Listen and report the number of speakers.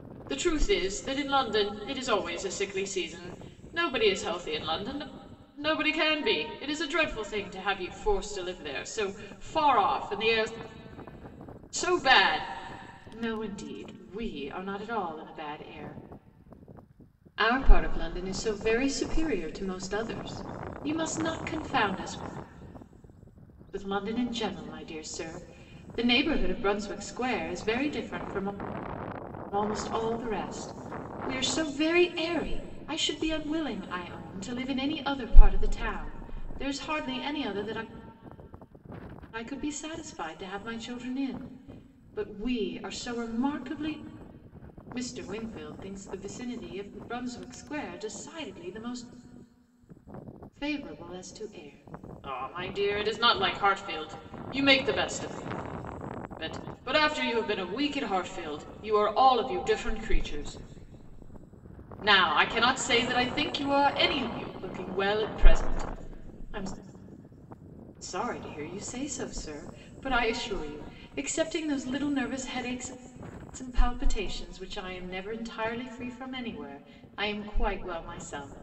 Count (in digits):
1